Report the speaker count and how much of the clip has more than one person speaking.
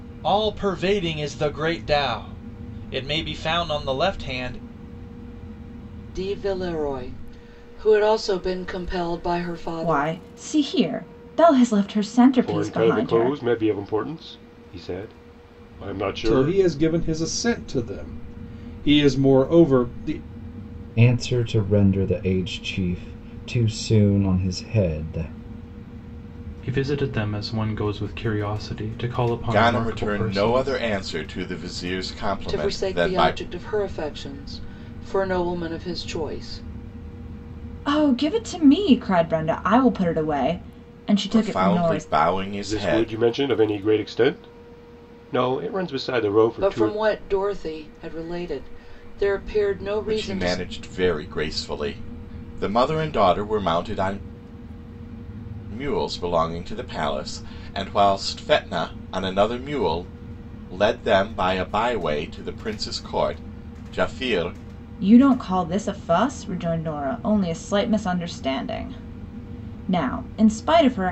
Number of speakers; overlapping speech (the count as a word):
eight, about 9%